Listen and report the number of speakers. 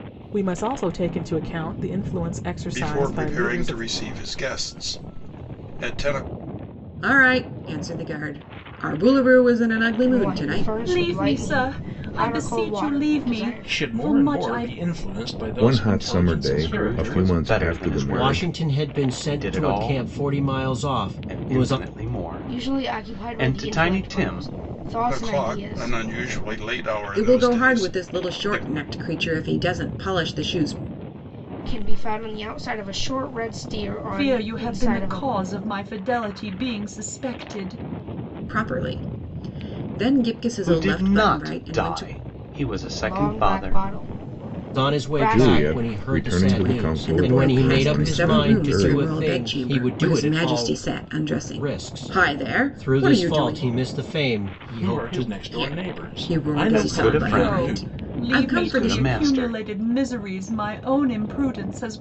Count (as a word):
nine